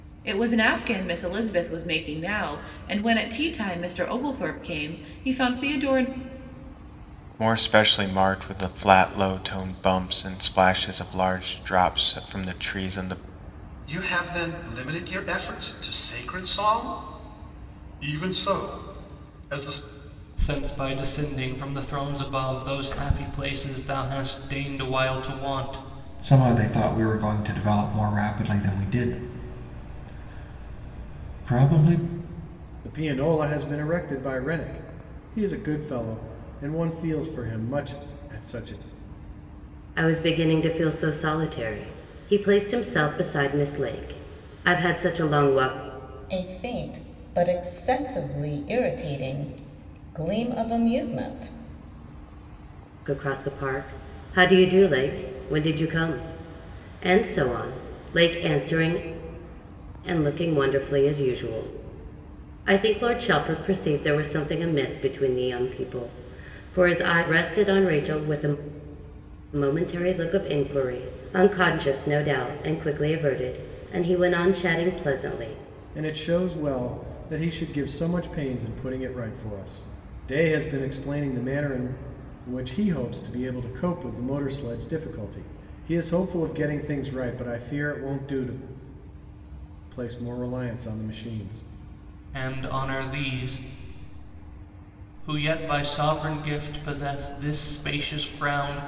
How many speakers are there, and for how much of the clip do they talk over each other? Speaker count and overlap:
8, no overlap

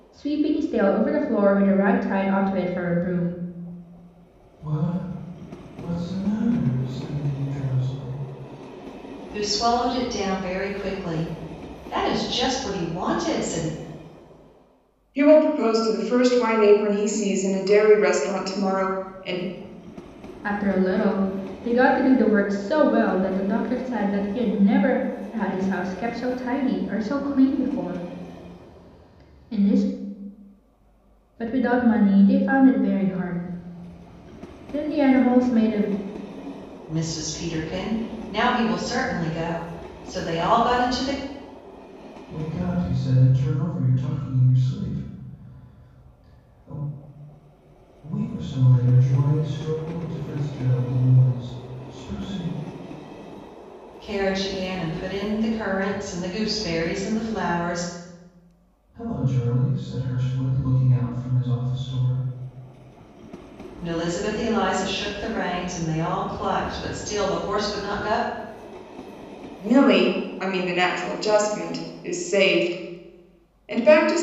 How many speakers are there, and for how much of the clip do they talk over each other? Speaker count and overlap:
4, no overlap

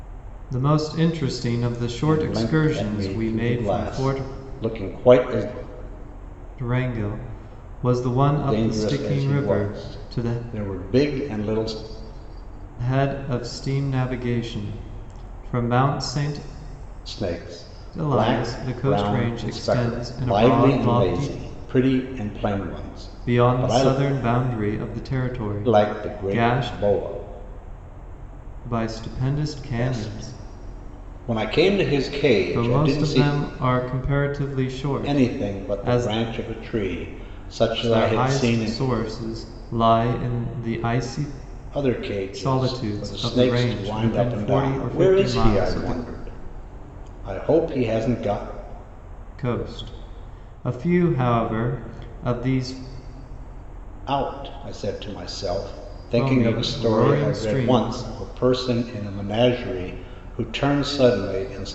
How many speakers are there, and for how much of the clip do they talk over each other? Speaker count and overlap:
2, about 31%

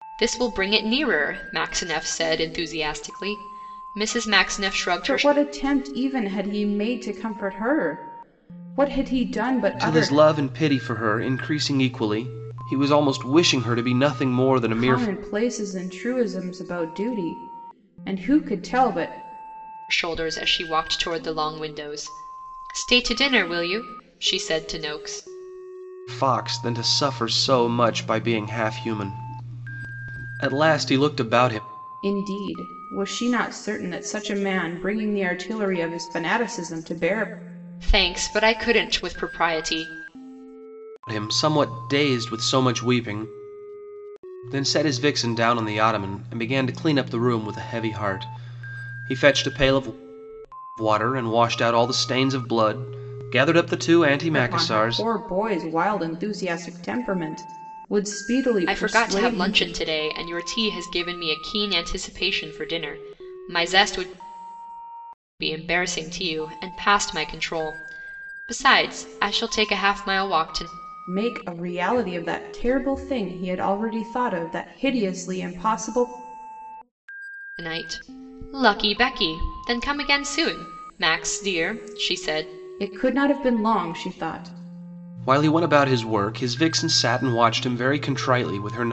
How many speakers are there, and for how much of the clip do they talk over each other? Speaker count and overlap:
3, about 3%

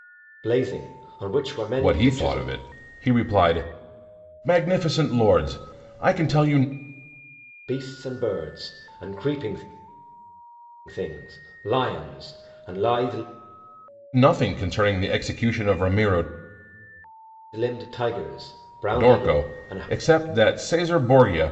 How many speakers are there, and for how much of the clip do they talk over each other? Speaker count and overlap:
2, about 8%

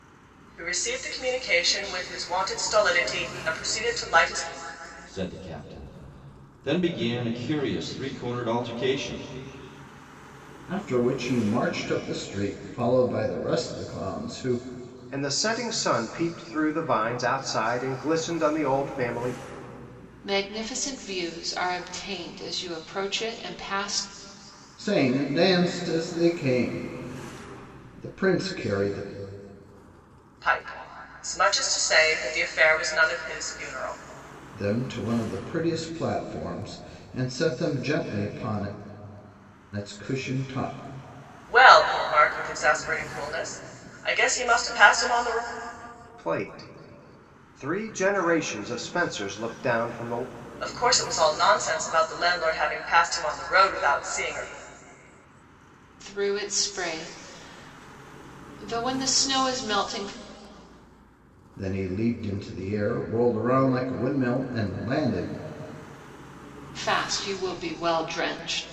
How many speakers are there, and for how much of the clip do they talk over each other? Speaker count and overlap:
5, no overlap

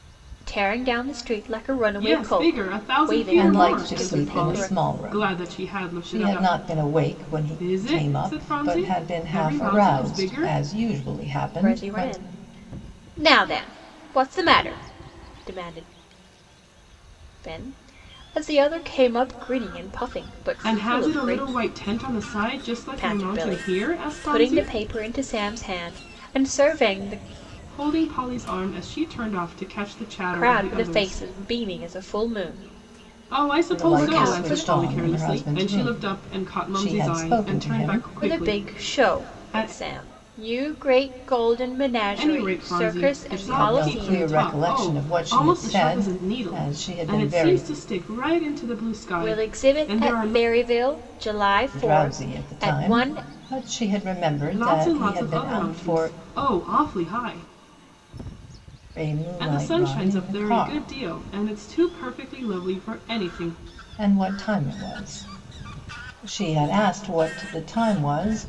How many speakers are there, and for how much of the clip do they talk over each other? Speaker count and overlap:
3, about 44%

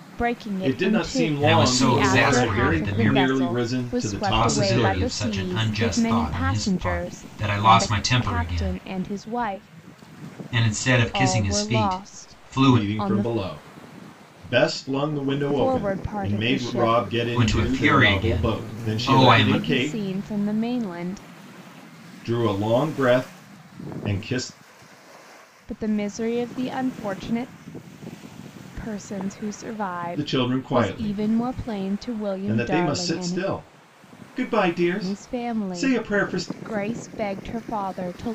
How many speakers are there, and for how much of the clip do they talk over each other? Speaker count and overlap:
3, about 46%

